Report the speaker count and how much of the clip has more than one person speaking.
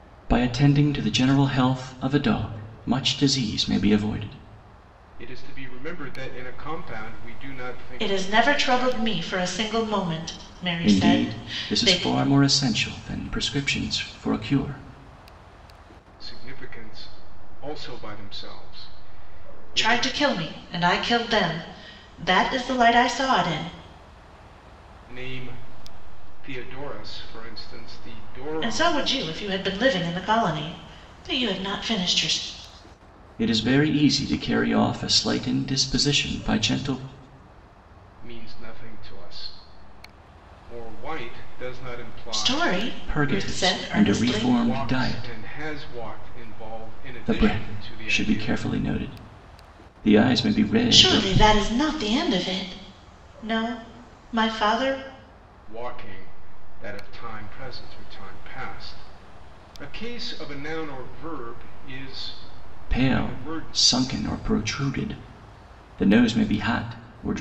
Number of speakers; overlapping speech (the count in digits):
3, about 13%